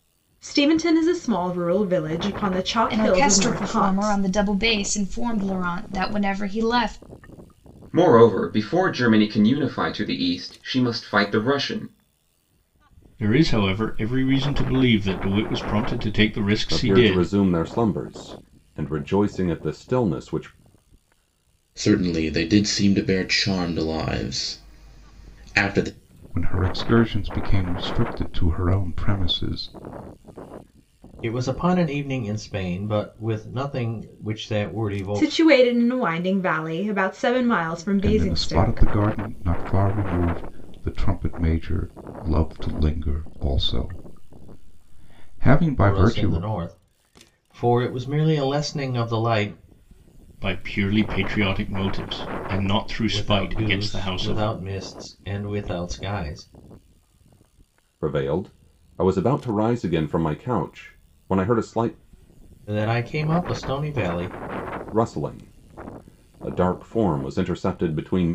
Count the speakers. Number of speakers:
8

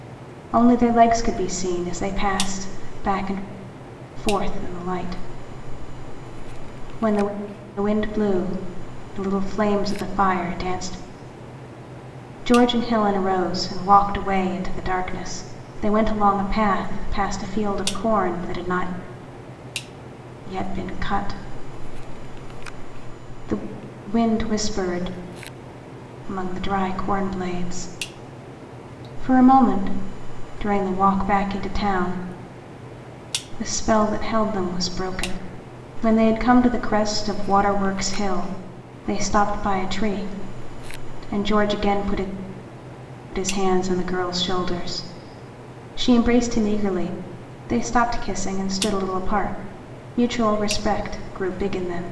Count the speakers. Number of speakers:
1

